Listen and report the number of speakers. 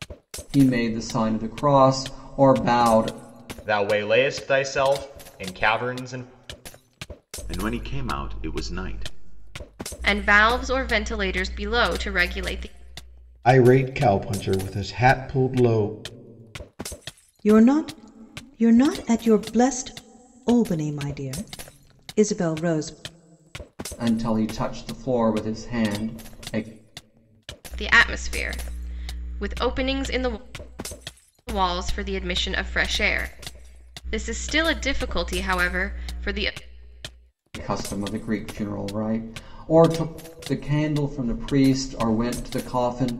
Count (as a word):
six